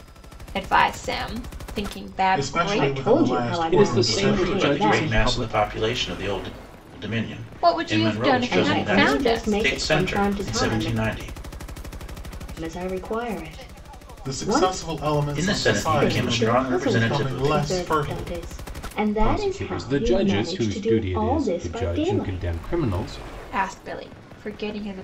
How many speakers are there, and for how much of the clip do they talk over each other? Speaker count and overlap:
5, about 55%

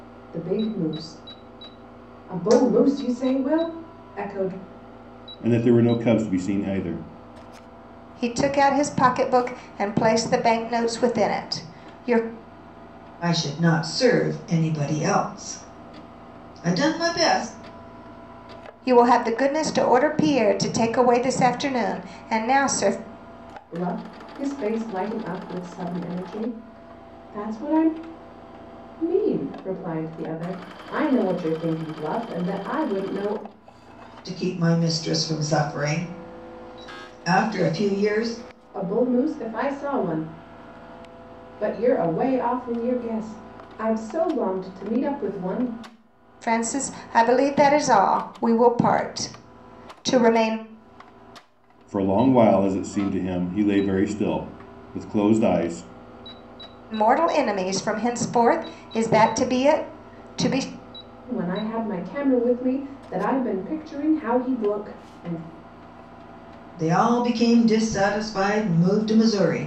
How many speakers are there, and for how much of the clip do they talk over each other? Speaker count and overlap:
4, no overlap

